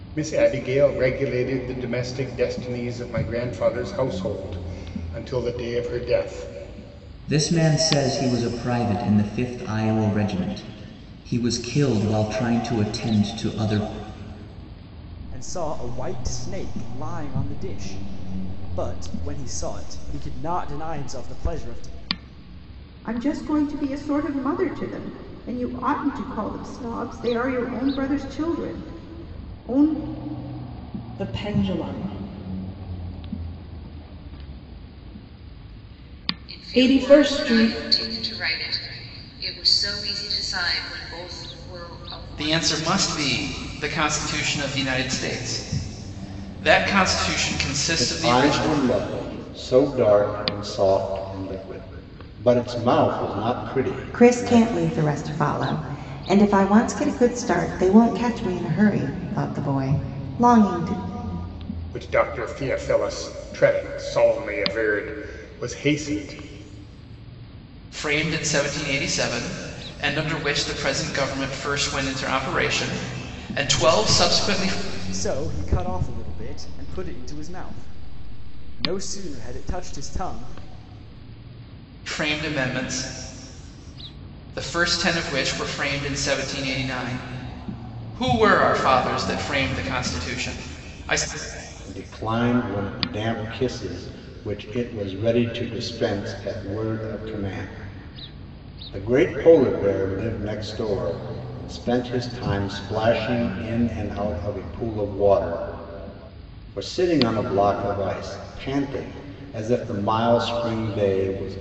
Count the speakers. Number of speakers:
nine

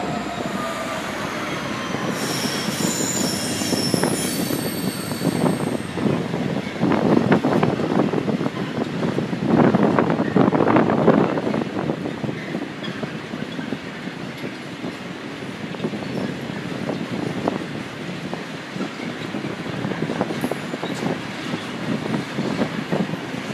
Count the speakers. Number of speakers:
zero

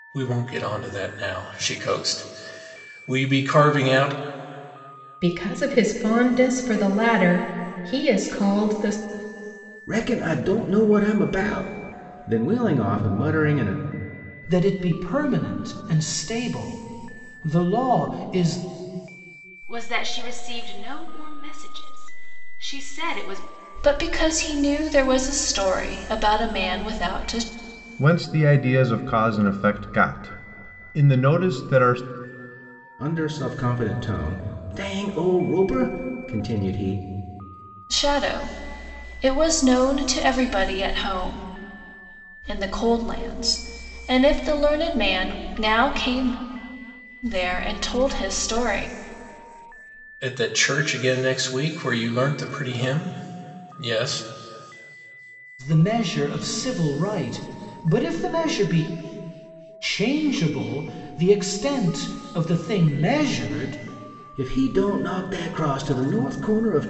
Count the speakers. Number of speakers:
seven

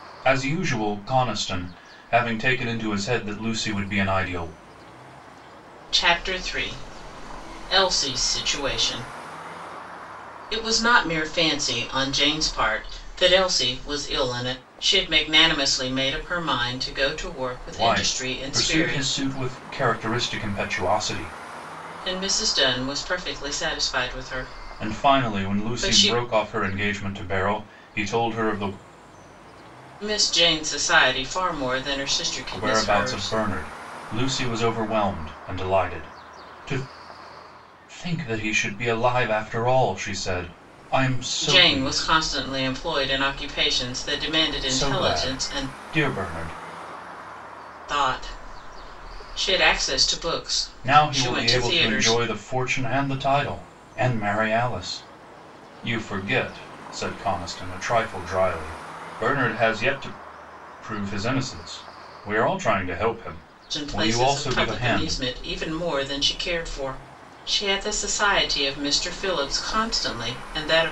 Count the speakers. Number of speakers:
two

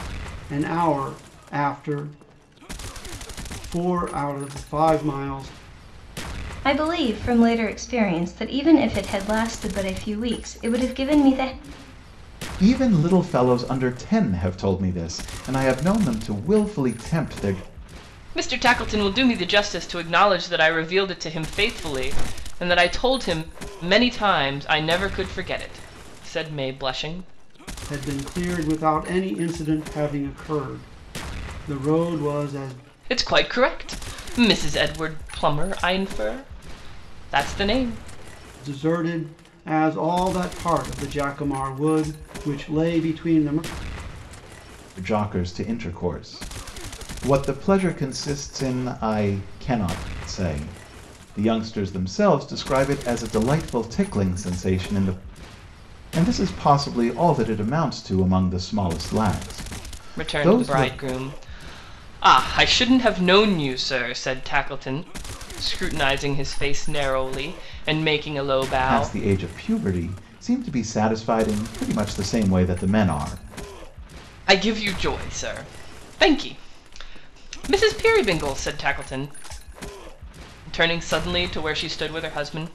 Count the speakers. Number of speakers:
four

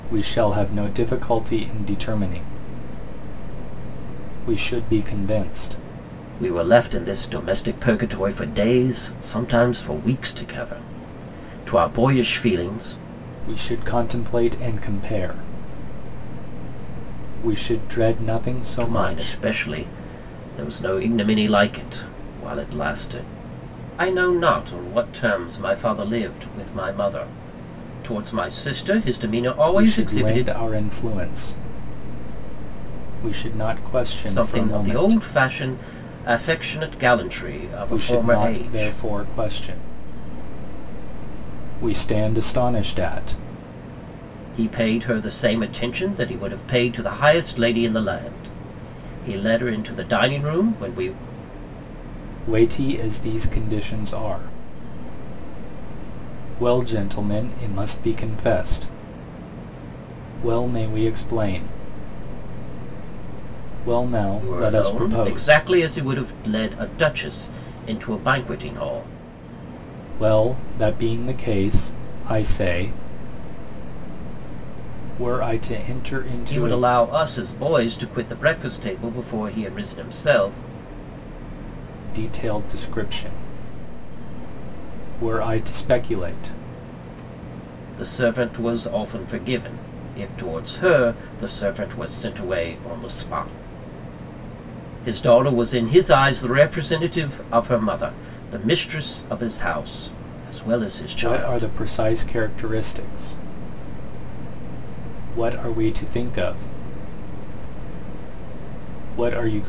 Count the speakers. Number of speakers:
two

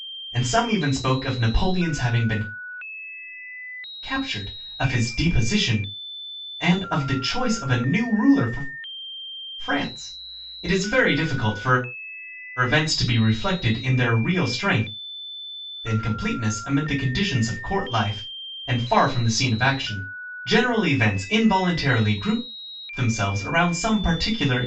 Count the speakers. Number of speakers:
one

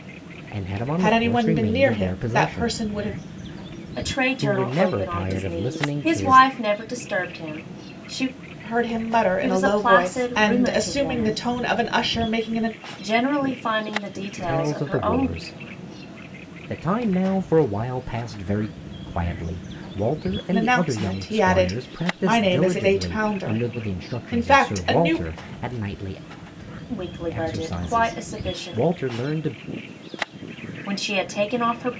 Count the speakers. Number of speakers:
three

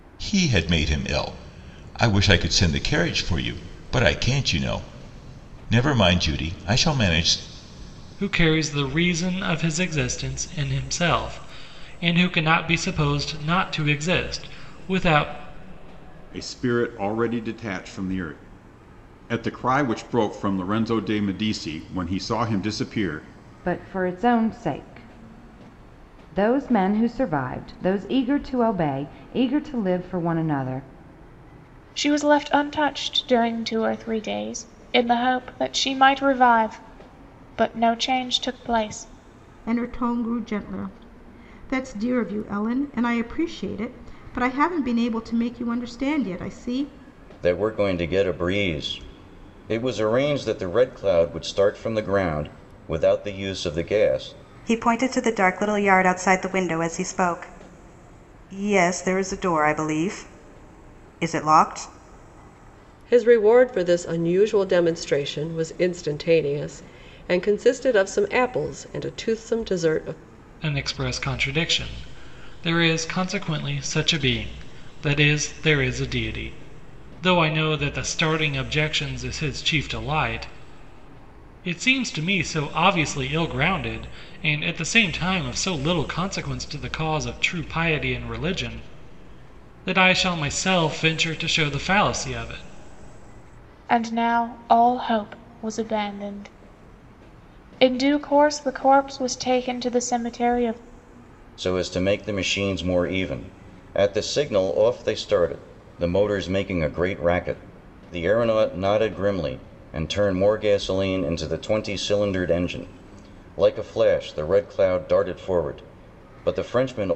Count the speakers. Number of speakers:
nine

